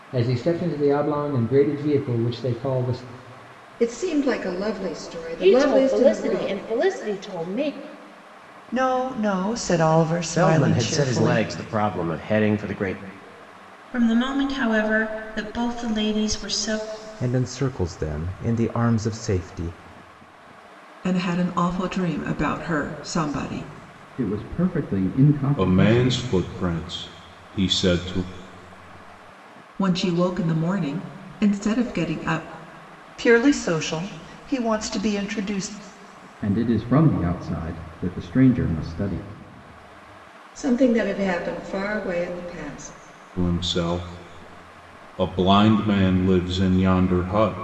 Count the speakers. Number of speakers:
ten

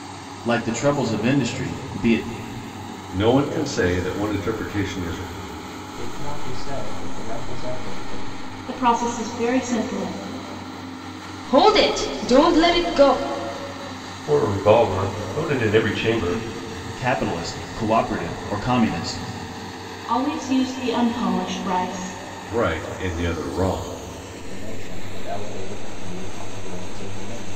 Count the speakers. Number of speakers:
six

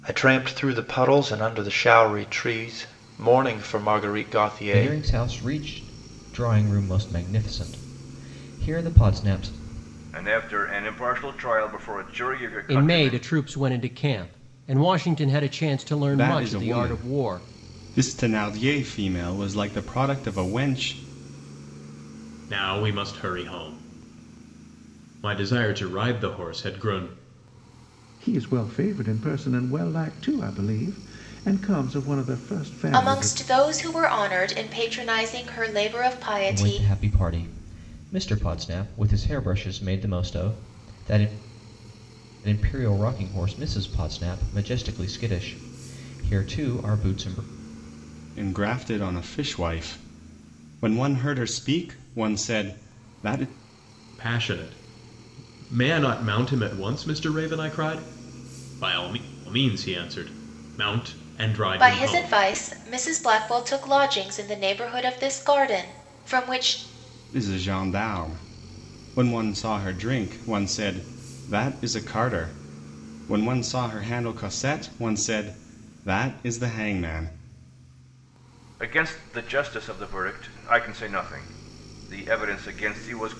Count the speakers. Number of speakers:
eight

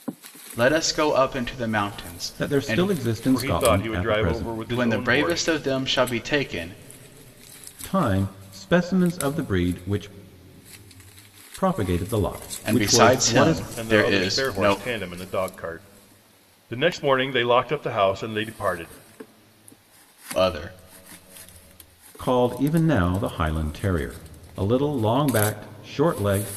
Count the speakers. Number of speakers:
three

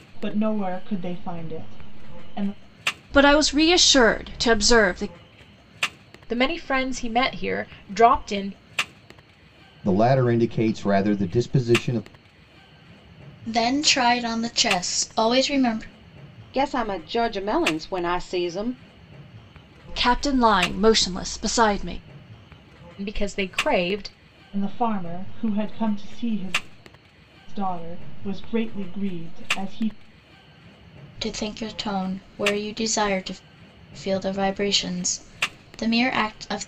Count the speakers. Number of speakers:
six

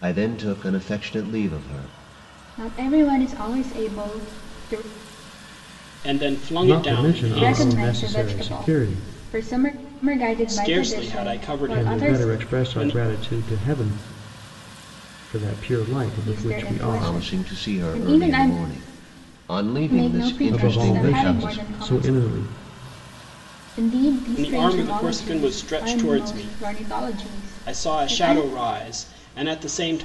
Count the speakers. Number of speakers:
four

